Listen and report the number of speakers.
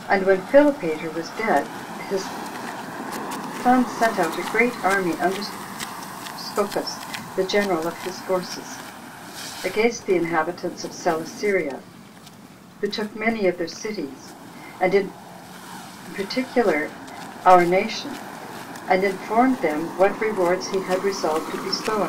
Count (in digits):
1